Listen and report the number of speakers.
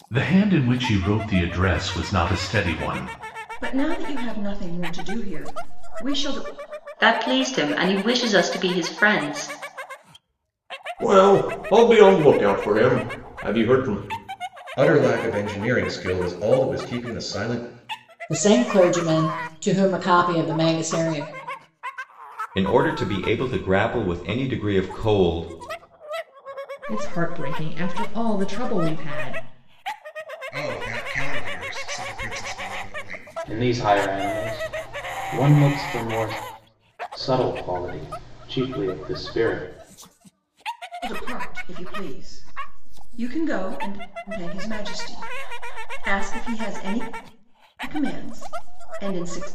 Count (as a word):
ten